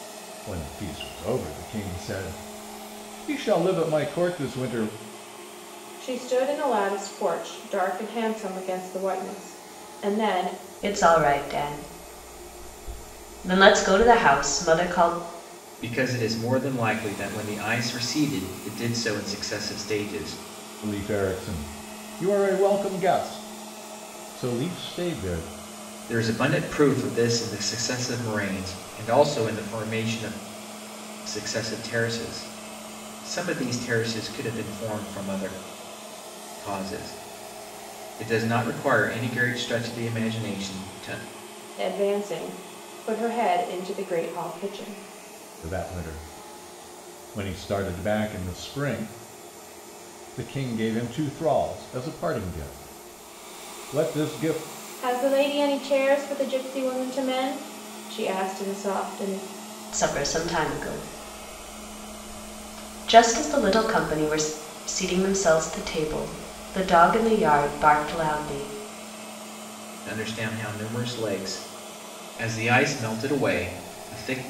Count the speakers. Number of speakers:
4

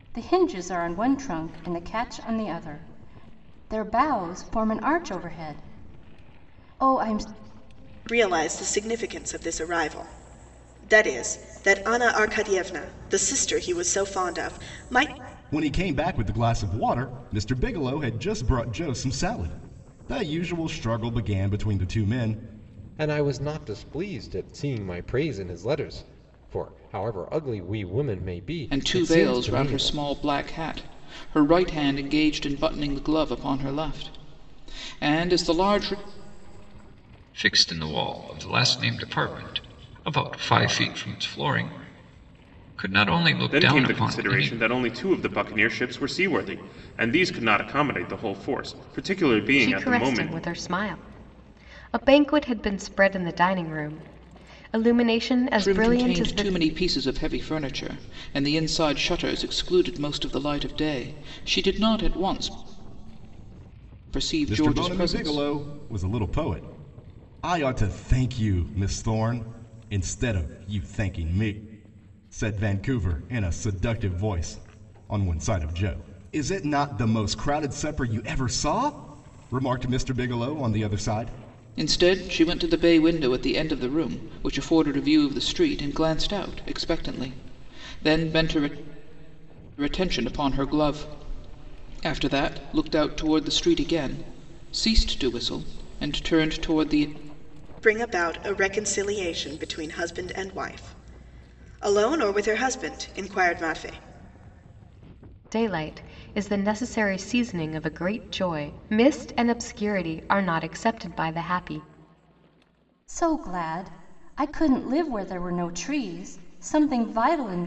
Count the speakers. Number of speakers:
8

